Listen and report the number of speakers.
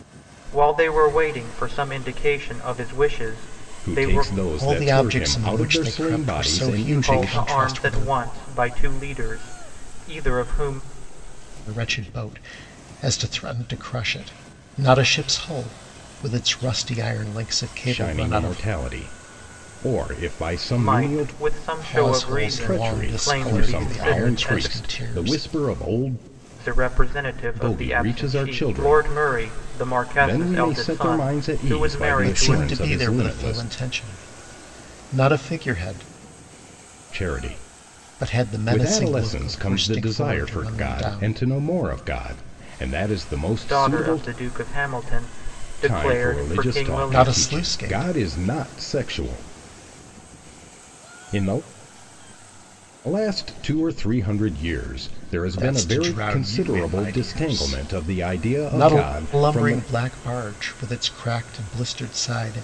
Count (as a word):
three